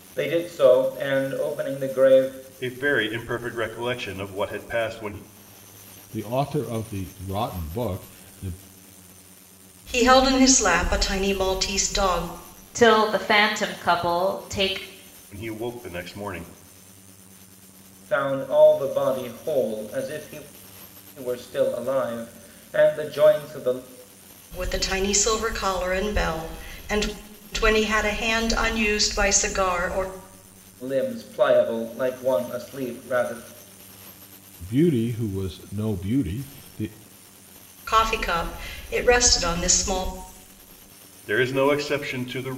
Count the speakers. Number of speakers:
5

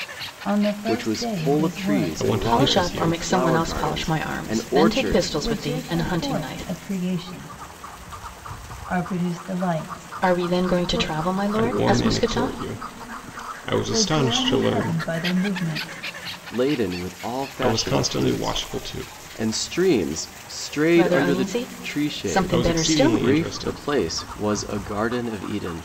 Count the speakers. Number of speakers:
4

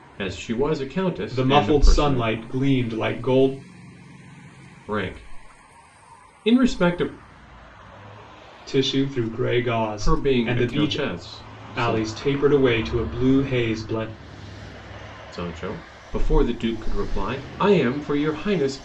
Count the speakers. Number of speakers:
2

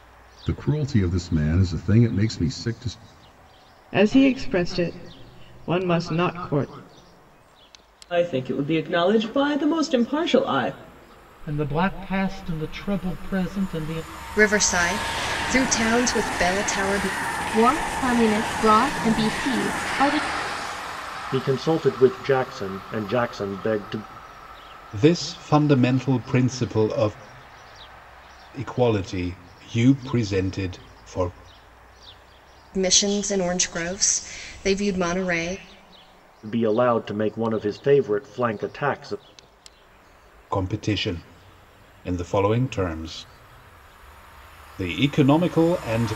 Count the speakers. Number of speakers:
8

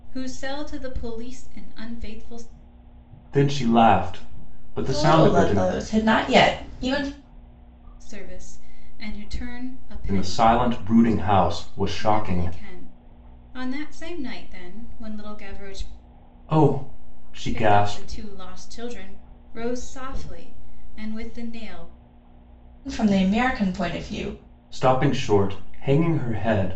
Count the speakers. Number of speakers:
3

